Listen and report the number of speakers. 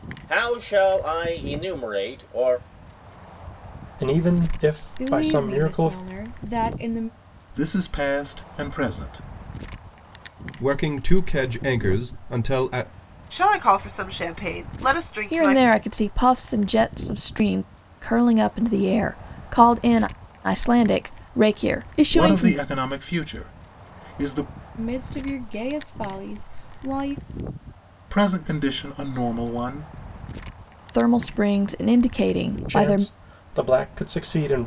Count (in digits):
7